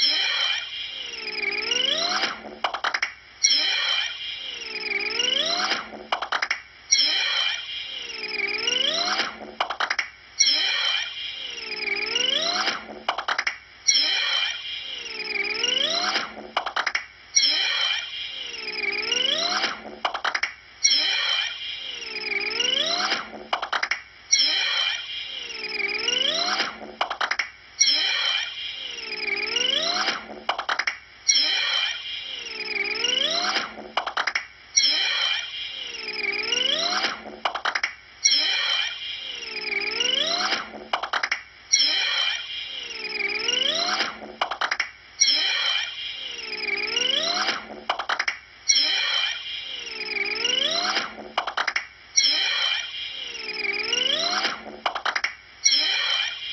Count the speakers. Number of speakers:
0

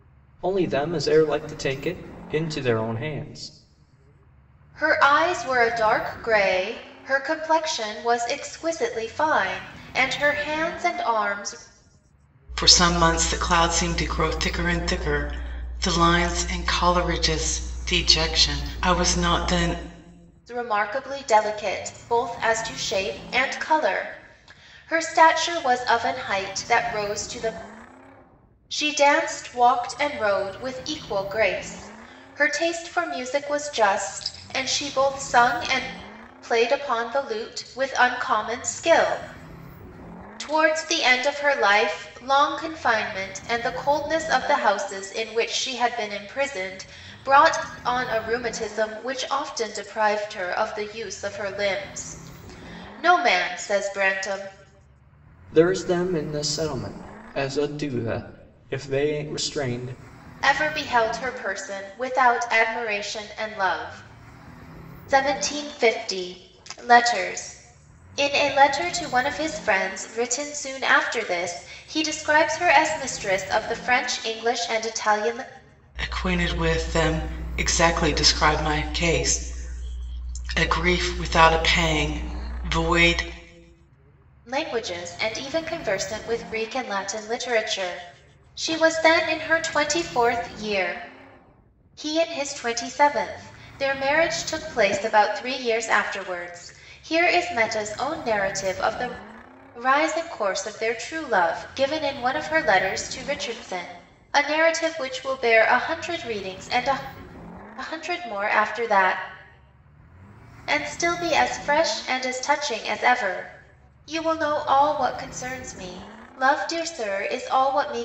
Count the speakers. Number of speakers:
3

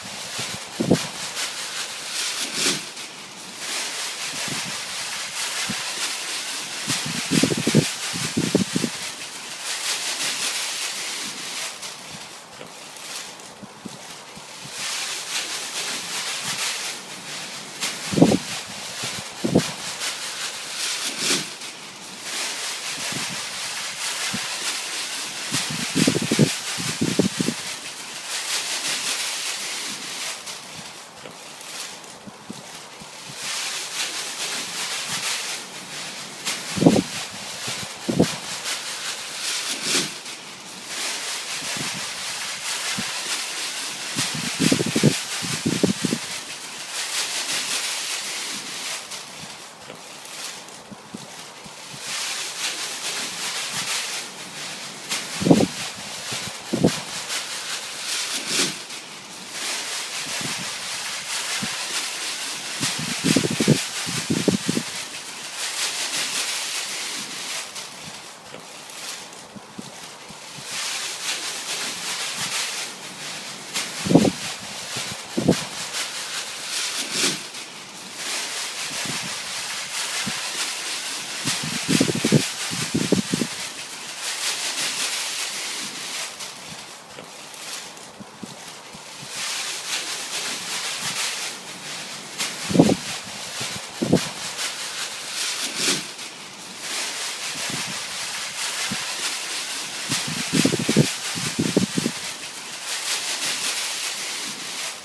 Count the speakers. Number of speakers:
0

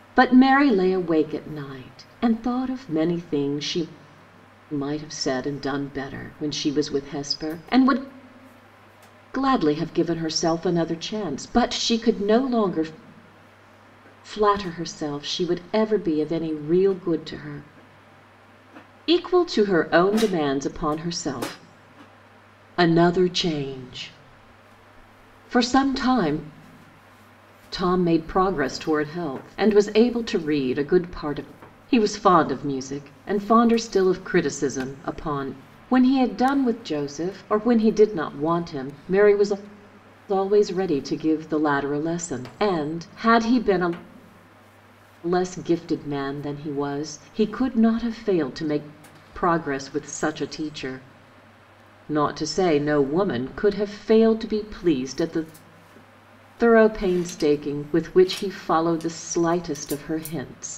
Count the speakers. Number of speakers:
1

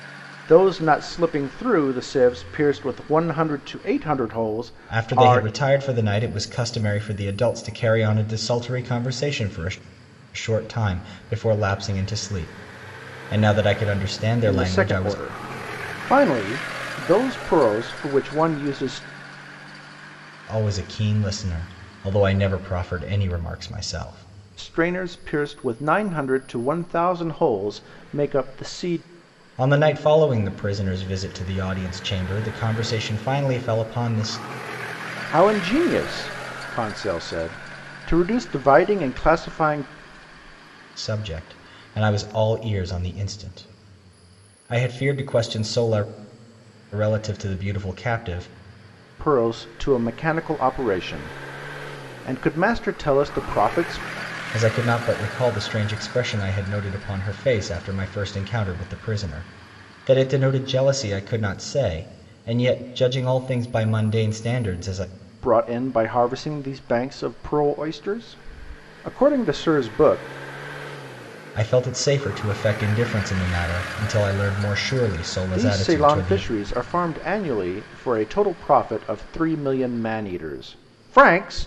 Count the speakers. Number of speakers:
2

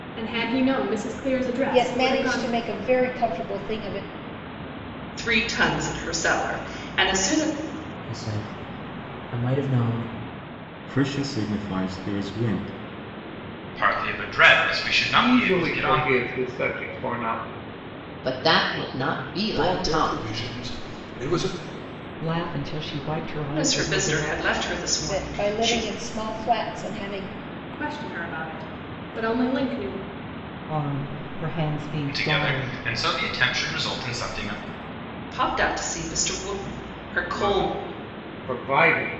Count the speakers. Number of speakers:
10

